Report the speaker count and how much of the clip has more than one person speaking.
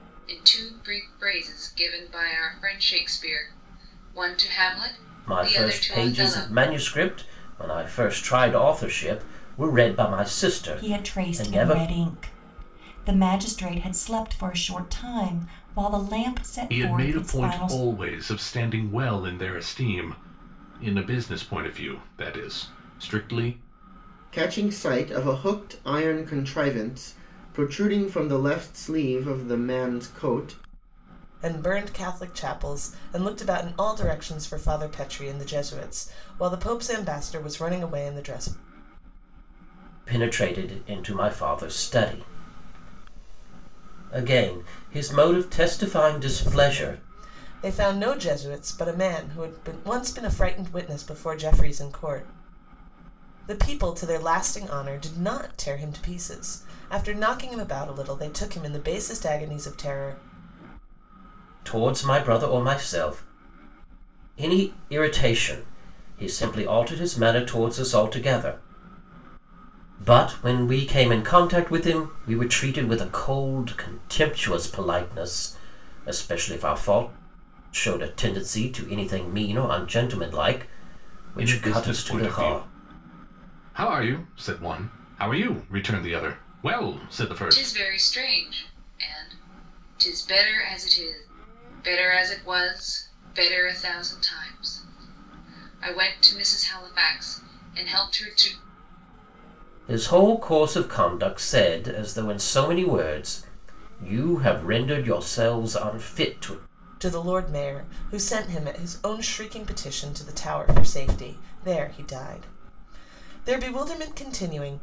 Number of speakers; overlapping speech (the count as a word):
six, about 5%